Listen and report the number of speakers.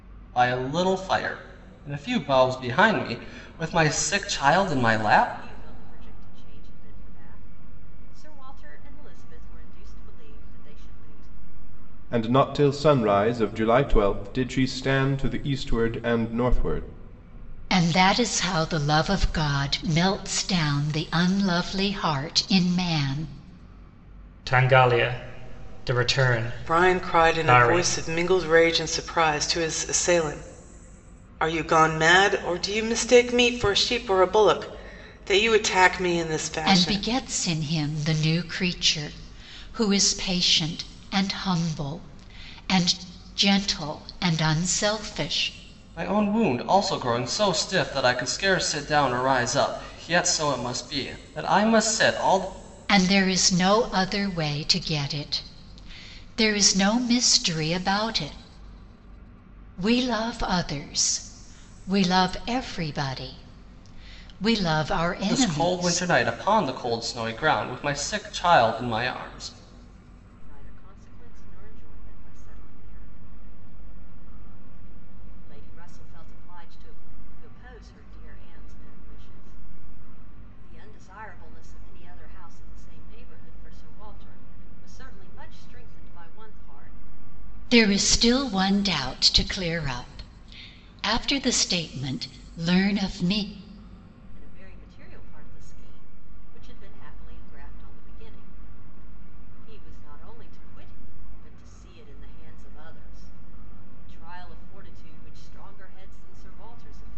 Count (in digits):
6